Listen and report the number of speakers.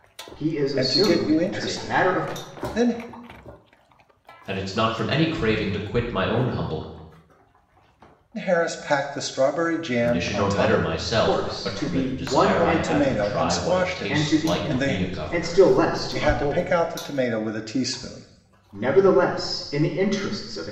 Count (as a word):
three